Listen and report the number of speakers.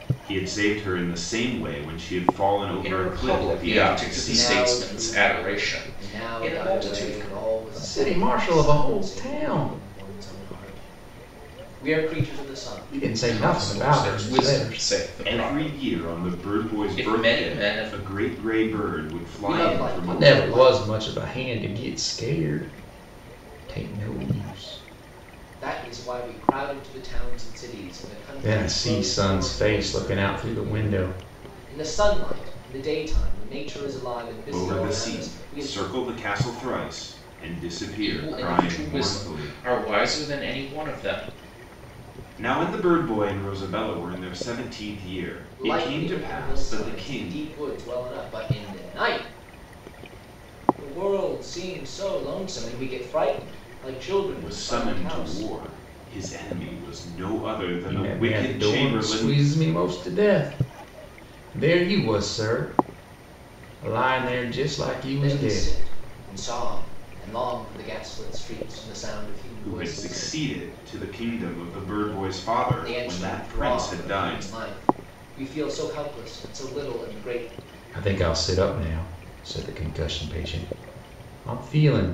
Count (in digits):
4